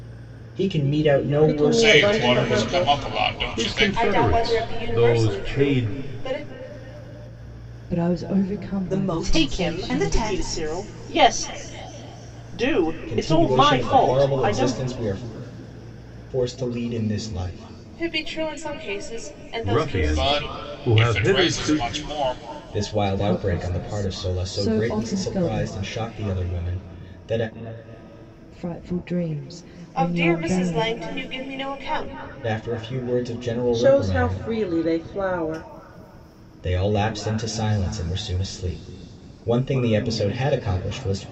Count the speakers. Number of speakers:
8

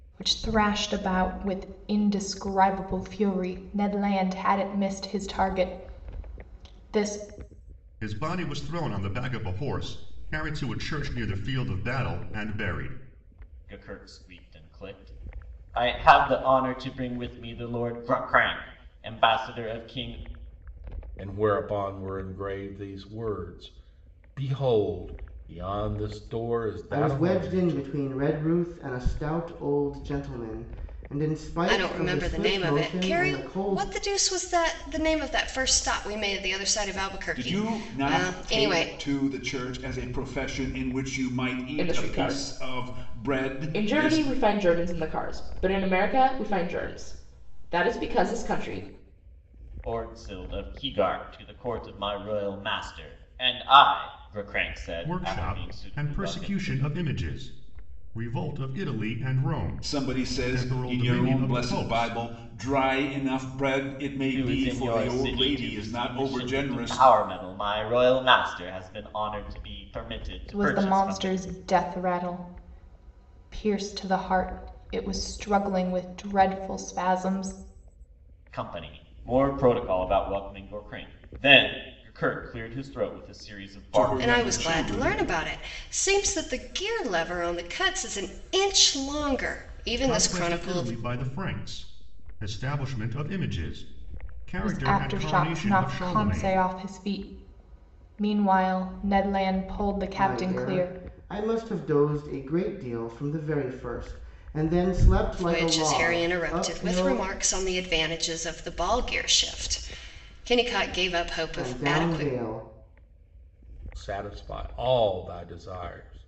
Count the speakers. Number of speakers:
8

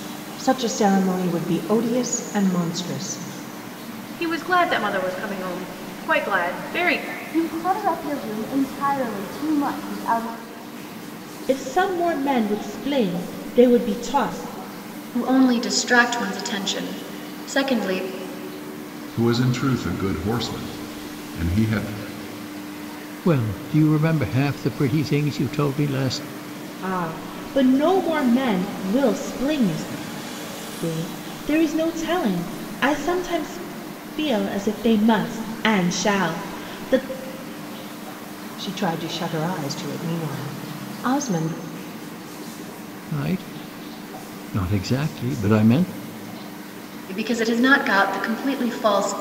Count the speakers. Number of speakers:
7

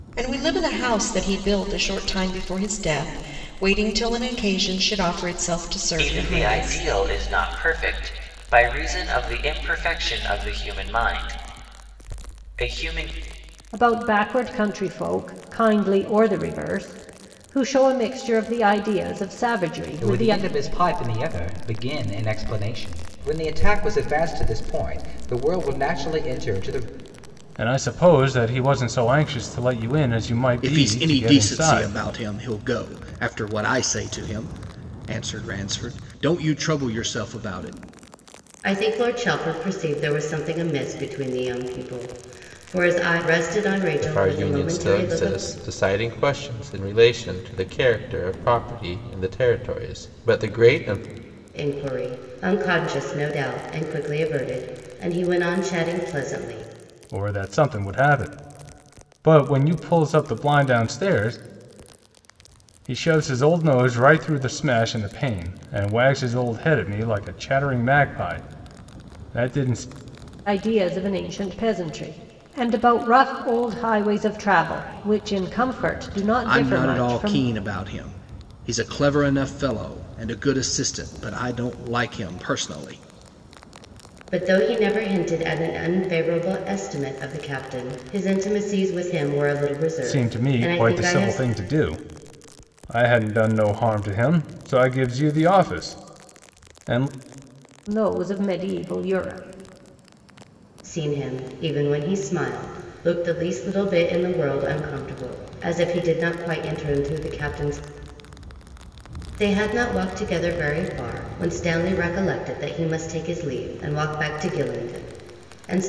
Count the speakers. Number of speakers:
8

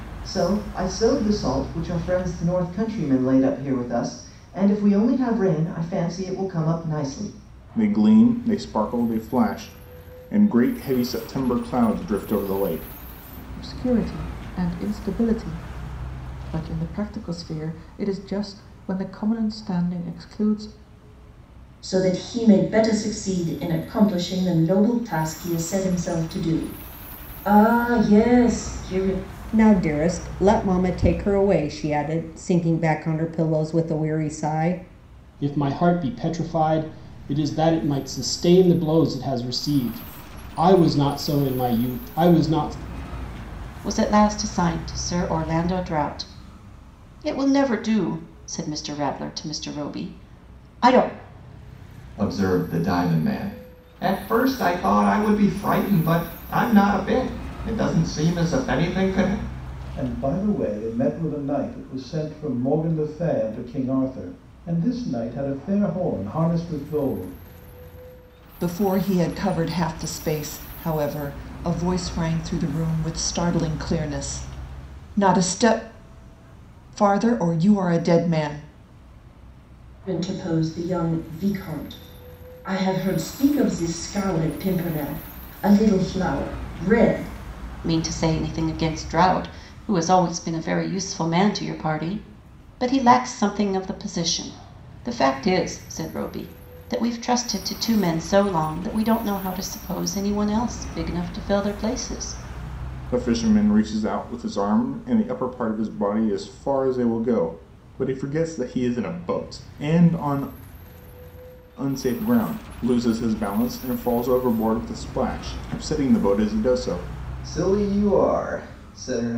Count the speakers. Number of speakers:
10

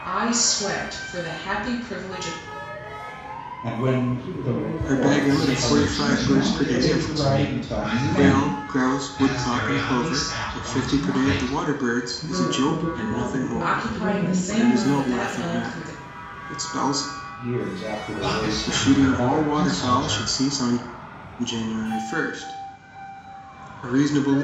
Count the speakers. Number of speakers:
5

